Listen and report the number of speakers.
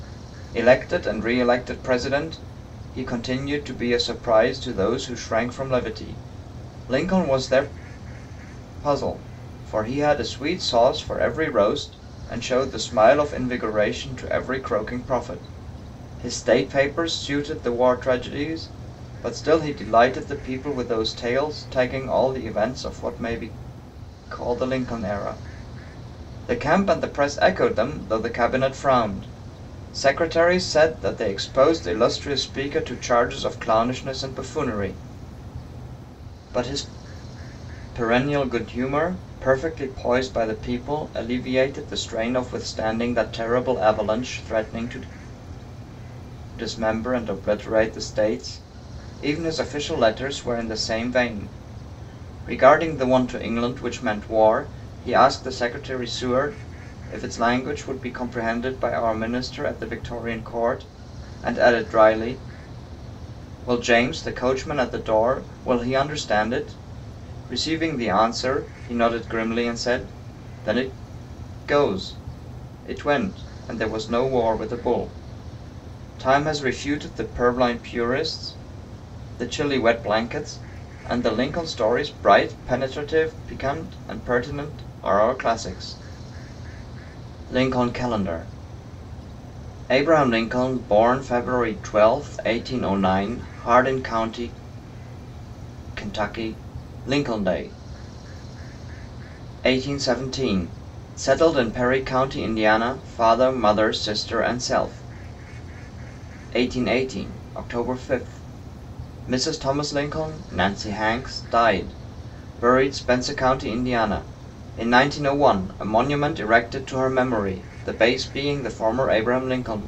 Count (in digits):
1